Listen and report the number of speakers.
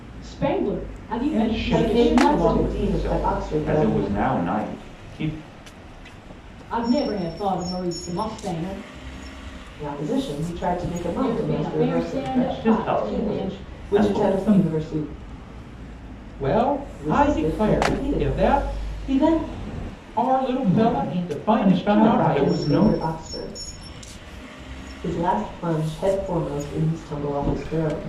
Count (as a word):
four